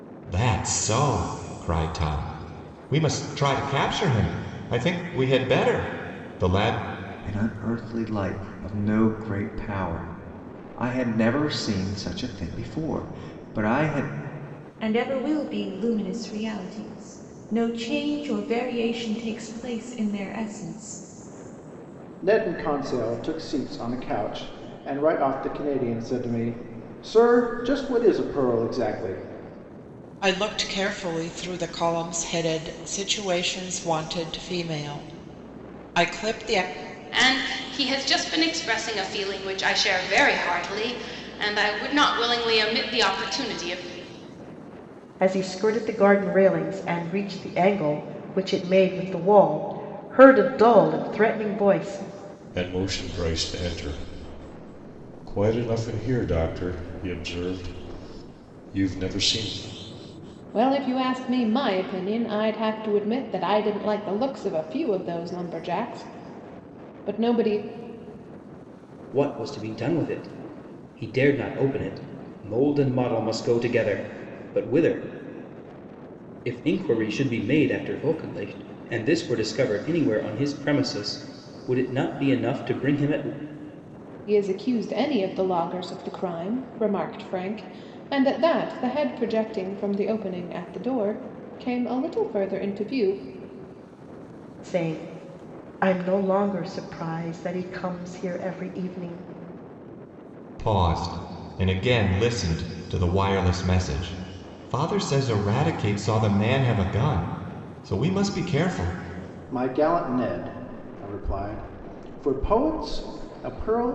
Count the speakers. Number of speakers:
10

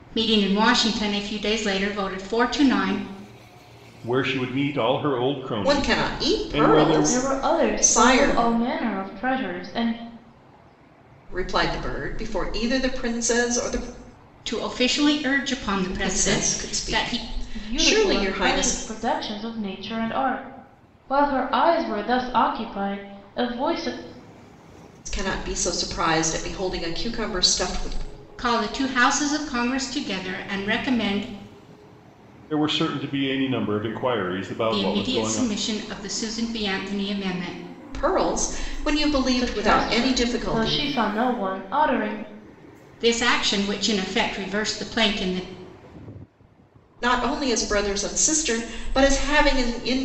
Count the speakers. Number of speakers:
4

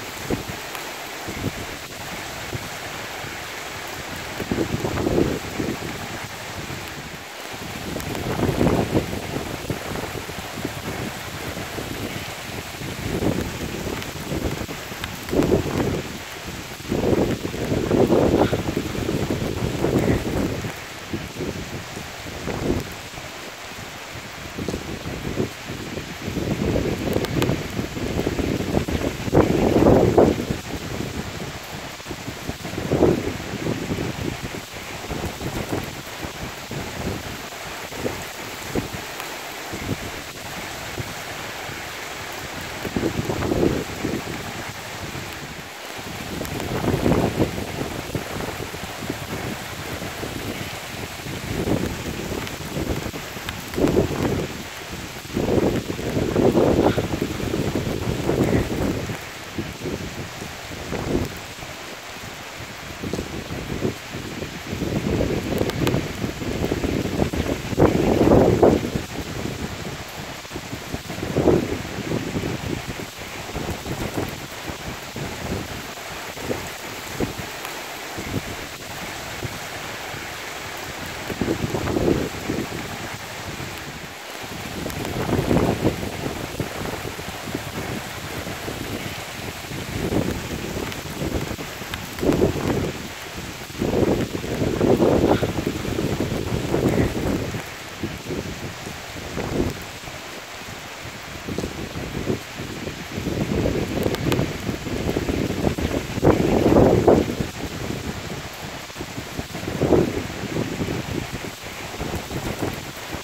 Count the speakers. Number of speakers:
0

